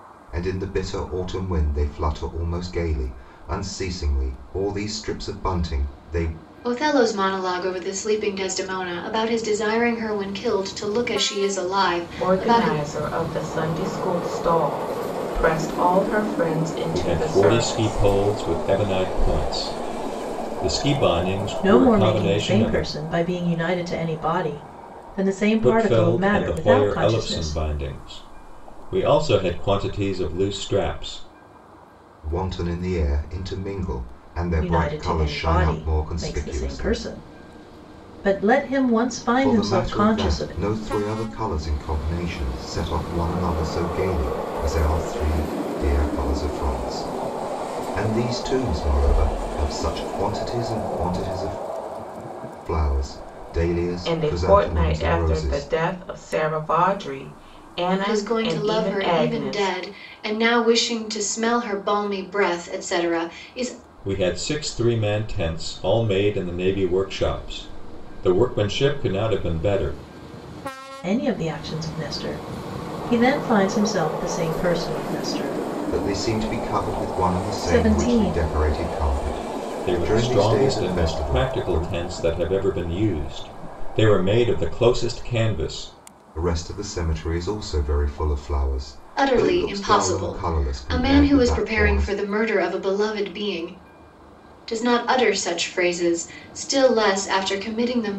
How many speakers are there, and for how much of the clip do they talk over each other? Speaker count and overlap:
5, about 20%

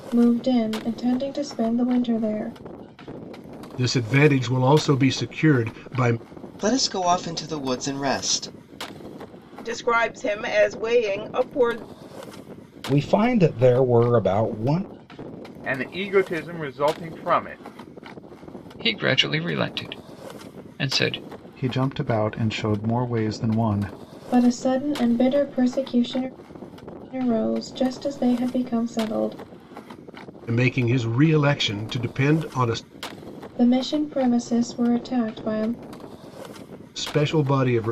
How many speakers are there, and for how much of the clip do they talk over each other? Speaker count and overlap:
8, no overlap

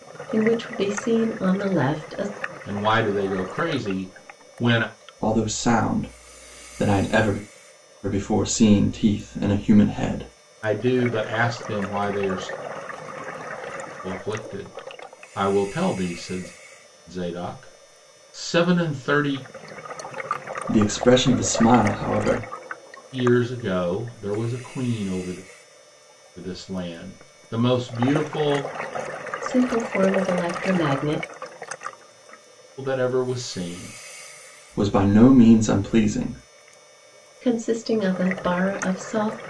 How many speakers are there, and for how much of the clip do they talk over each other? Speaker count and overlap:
3, no overlap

